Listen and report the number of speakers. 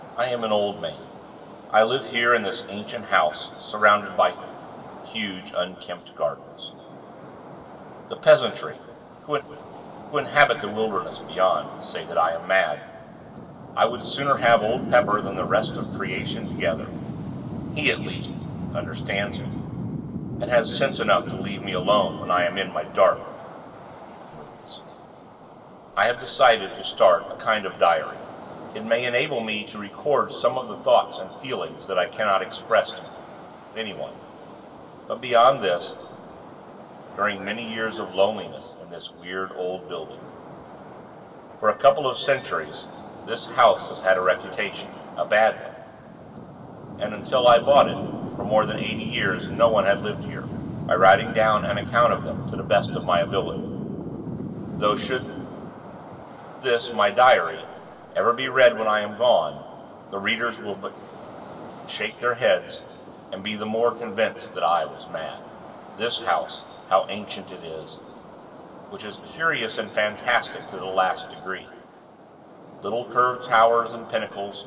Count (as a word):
one